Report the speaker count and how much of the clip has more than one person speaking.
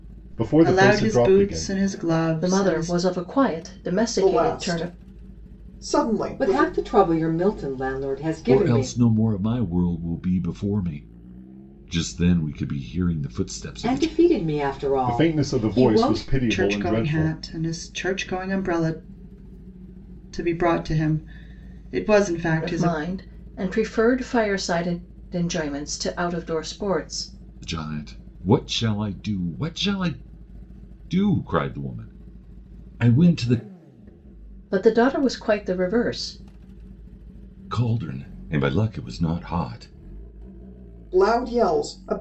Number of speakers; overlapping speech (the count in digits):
6, about 15%